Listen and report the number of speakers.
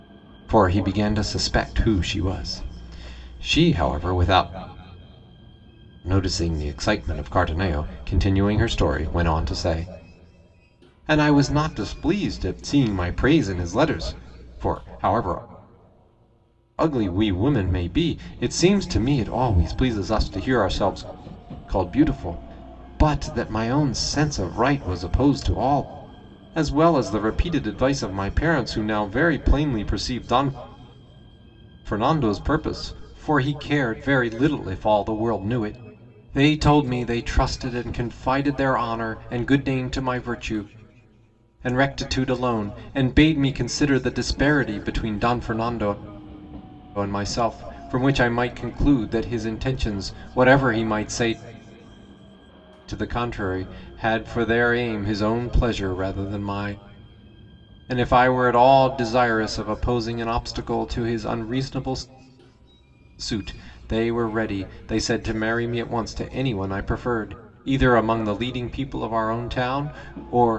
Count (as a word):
one